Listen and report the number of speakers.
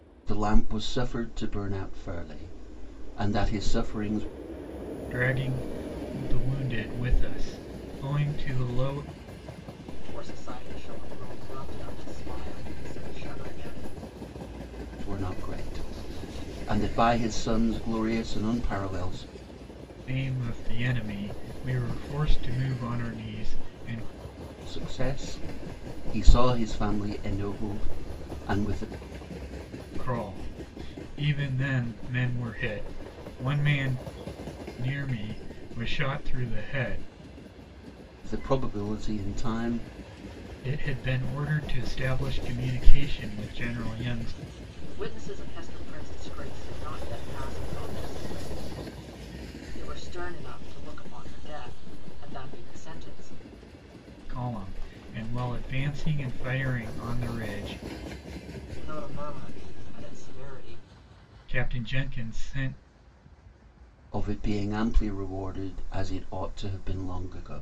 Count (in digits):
3